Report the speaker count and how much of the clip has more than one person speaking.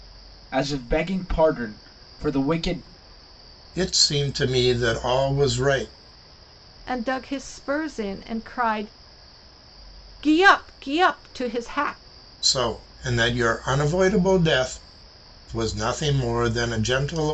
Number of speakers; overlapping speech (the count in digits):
3, no overlap